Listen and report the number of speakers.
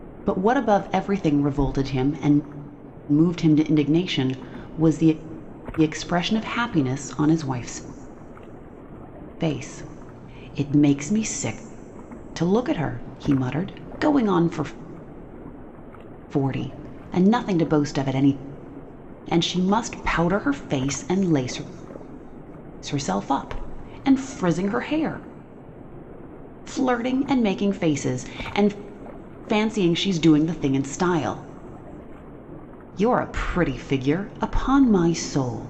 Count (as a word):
one